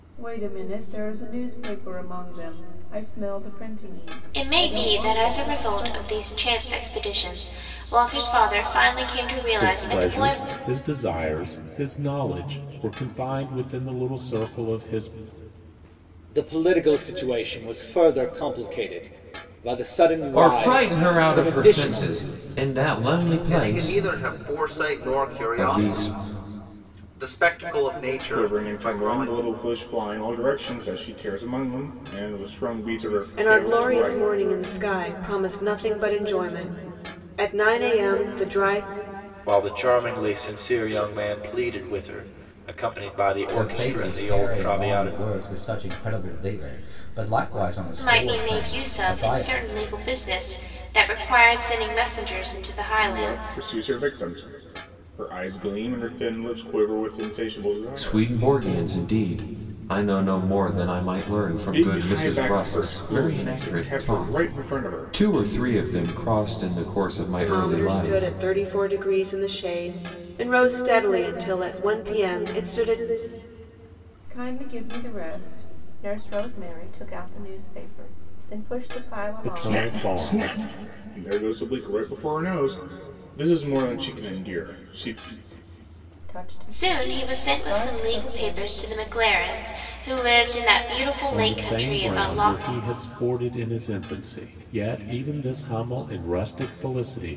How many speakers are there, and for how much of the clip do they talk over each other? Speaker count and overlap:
ten, about 24%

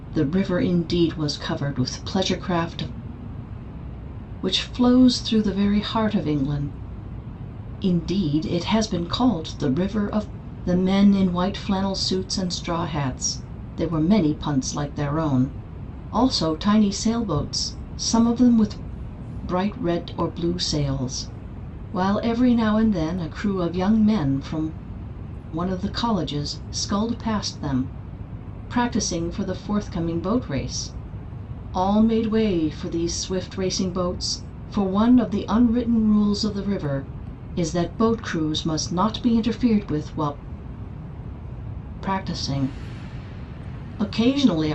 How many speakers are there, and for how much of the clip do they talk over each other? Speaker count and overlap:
one, no overlap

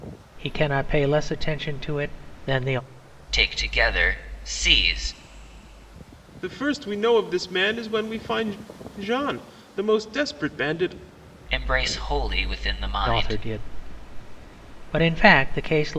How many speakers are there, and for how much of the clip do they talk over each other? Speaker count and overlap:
three, about 2%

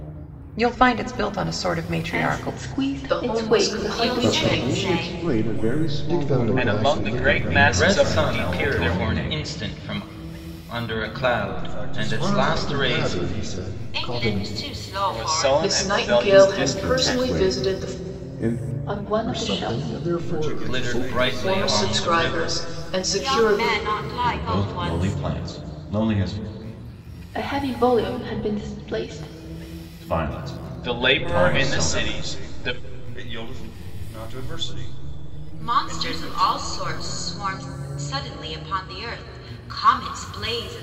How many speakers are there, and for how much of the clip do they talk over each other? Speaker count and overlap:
ten, about 50%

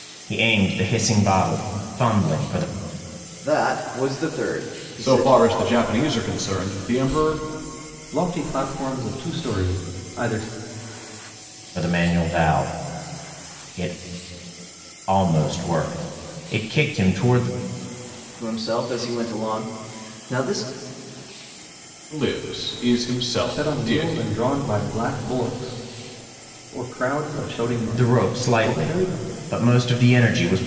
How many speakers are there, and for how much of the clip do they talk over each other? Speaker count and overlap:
four, about 8%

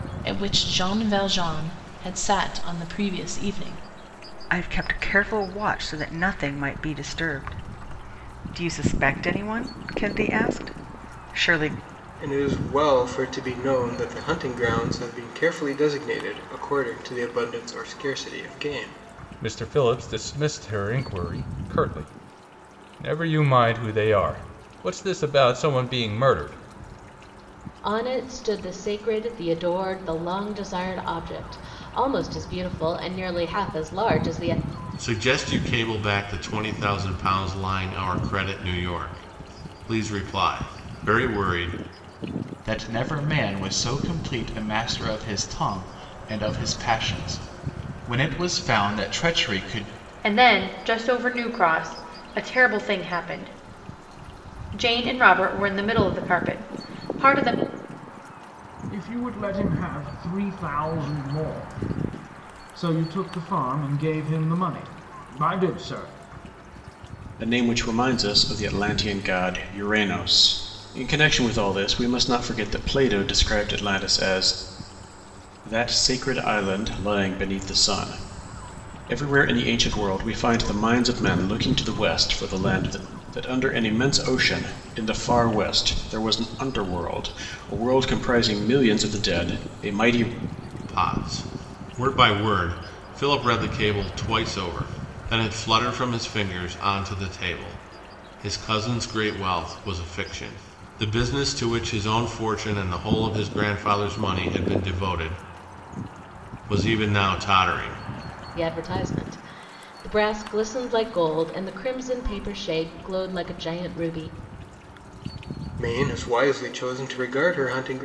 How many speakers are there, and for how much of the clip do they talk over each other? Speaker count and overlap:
ten, no overlap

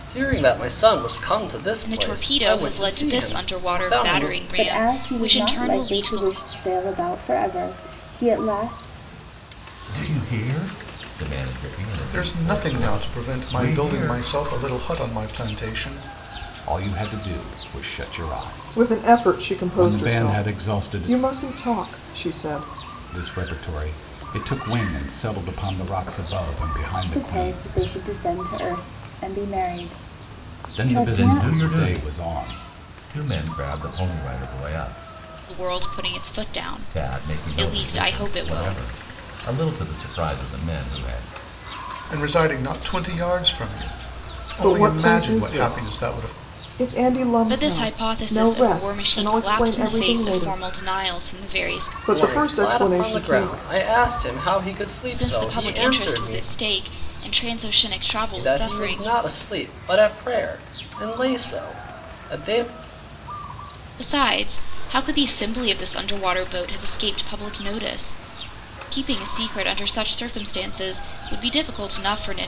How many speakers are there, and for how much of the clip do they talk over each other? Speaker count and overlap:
seven, about 32%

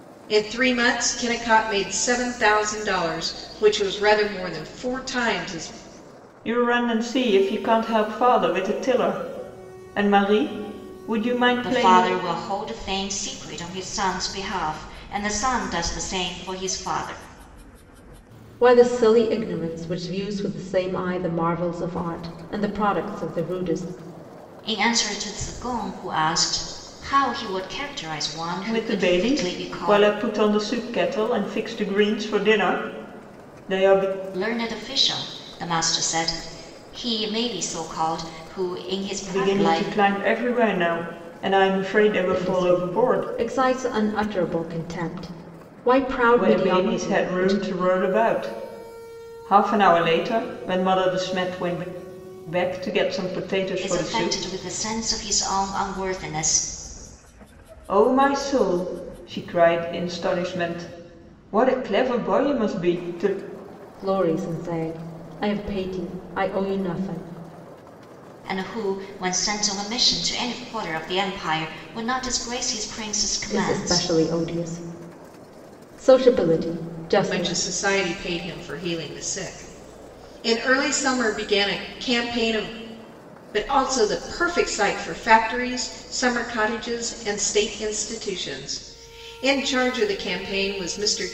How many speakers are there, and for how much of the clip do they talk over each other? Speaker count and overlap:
four, about 7%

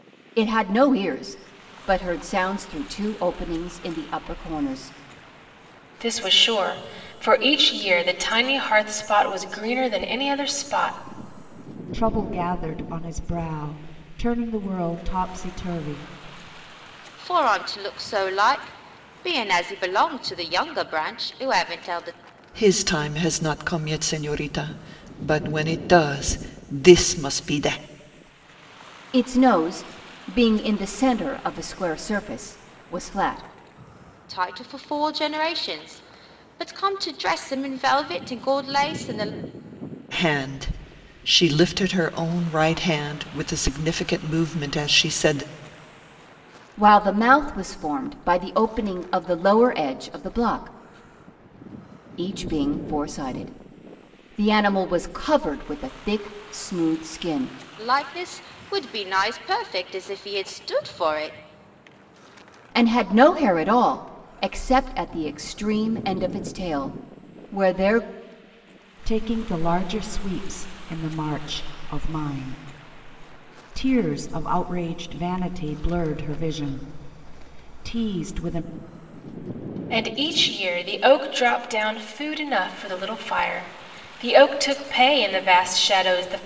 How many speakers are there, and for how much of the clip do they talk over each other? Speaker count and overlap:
five, no overlap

